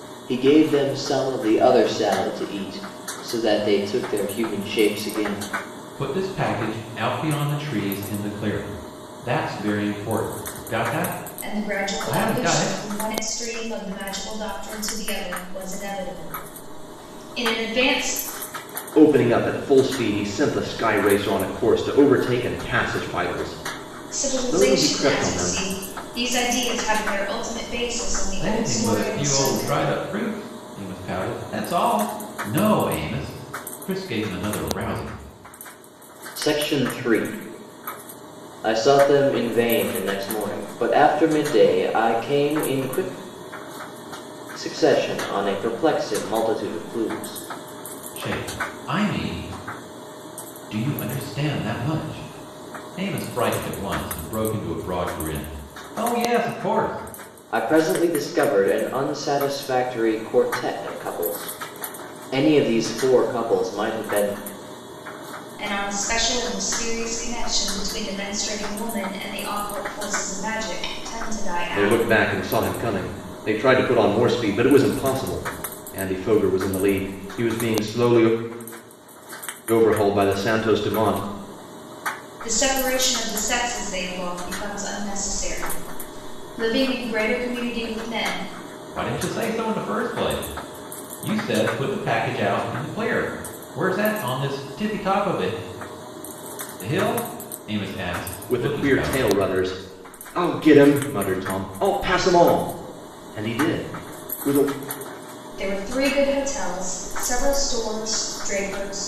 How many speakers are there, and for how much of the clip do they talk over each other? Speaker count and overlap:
four, about 5%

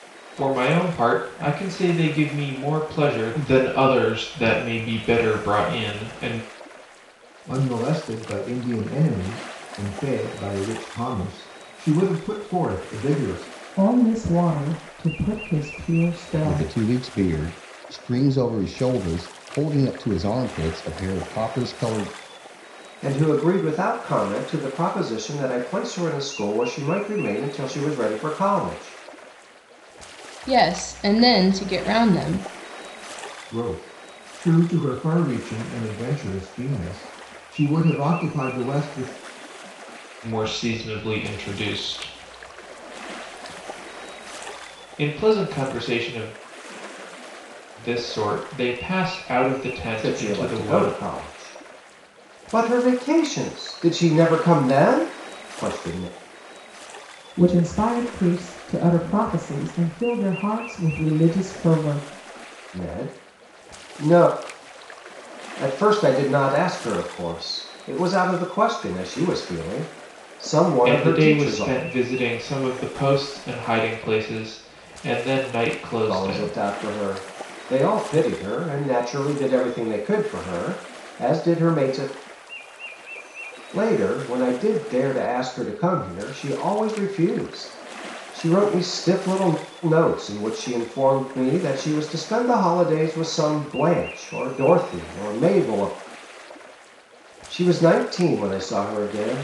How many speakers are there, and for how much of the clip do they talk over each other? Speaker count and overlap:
six, about 3%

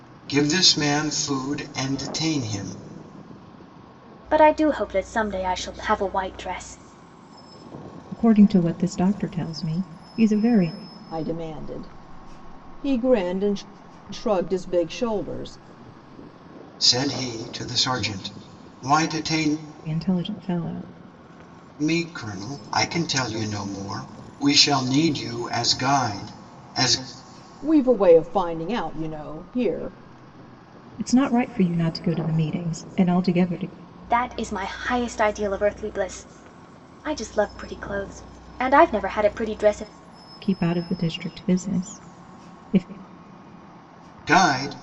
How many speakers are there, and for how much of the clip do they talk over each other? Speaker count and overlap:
four, no overlap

